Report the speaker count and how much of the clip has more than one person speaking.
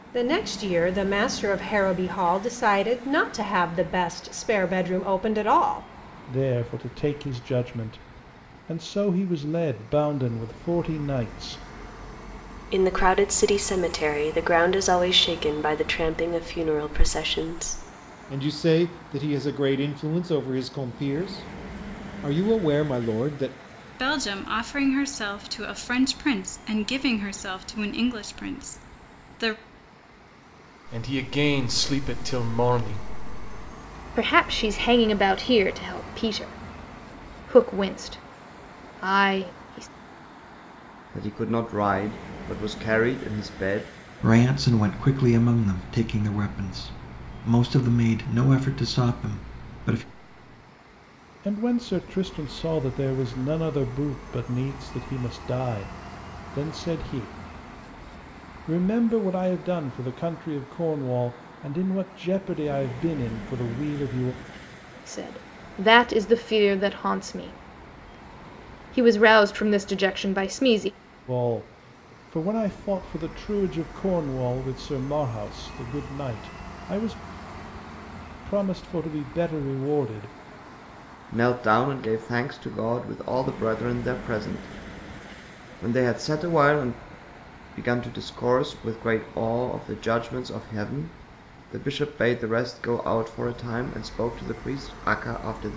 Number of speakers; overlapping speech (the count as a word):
nine, no overlap